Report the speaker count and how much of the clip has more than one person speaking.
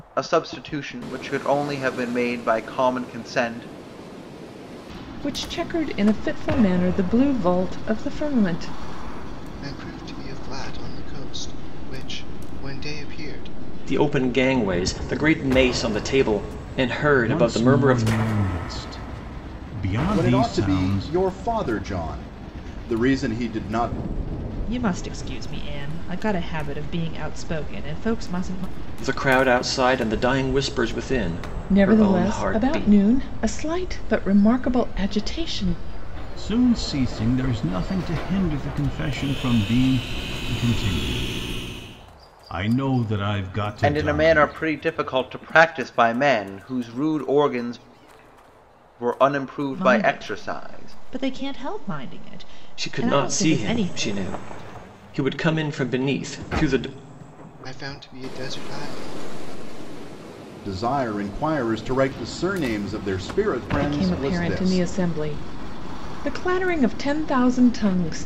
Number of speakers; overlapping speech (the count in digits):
7, about 11%